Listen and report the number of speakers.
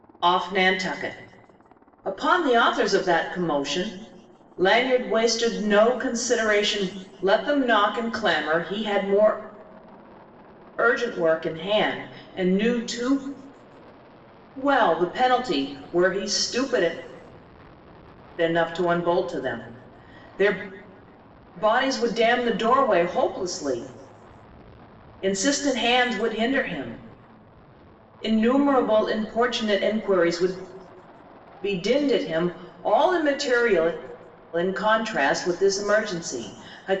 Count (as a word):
one